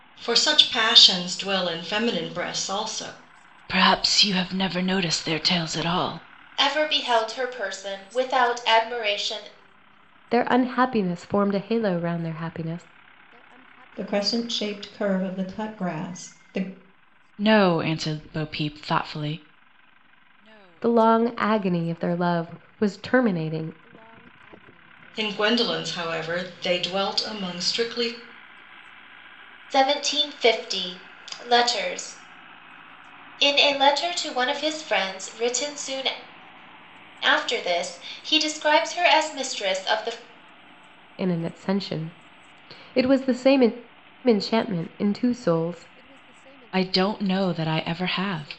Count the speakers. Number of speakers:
five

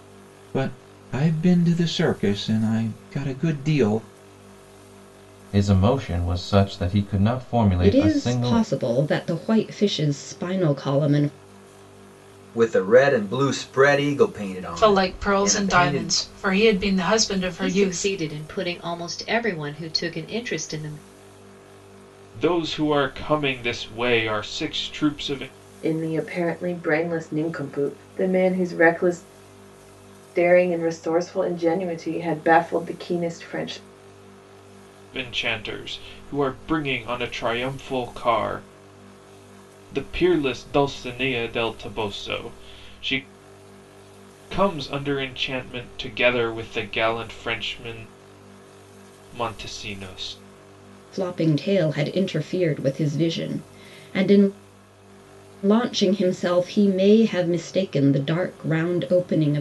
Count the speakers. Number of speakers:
eight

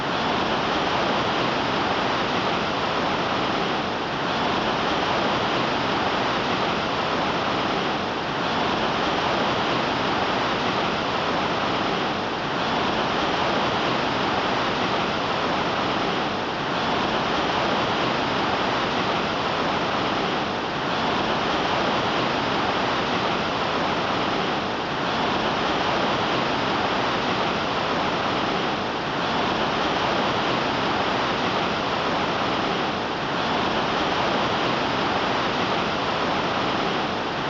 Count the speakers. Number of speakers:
zero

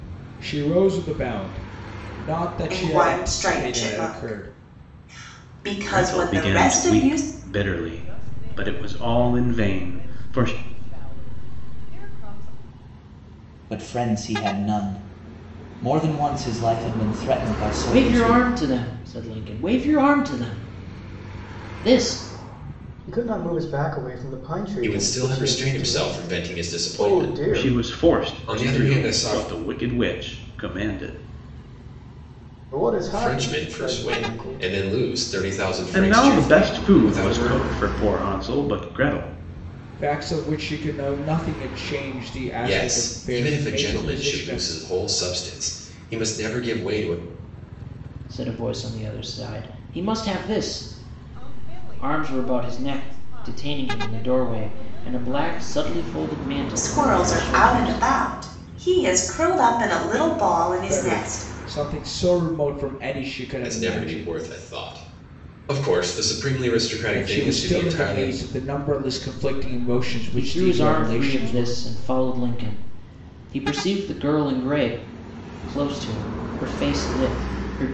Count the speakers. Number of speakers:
eight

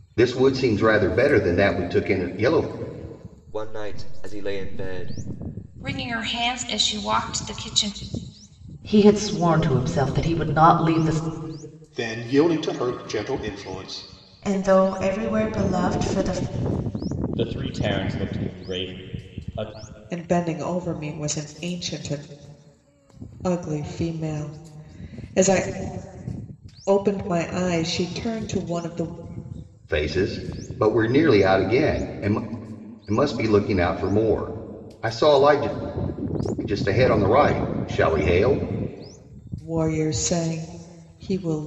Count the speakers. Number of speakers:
eight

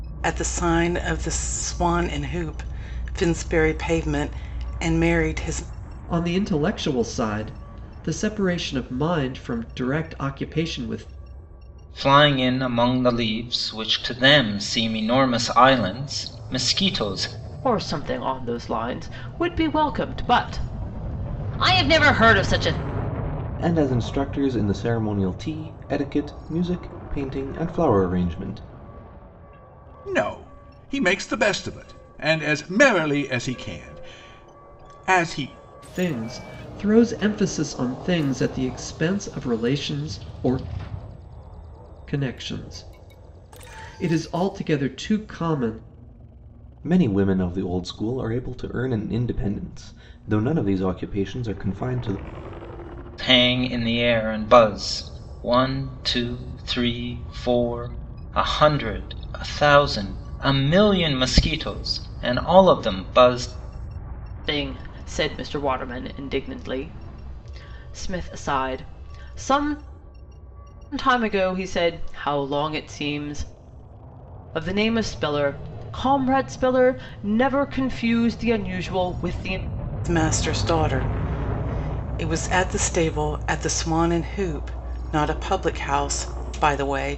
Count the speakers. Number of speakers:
six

